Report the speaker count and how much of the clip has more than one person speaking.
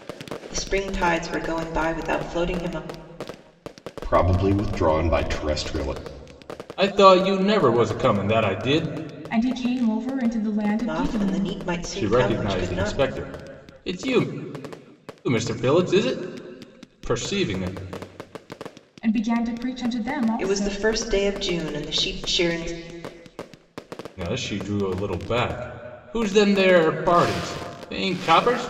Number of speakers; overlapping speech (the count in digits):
4, about 8%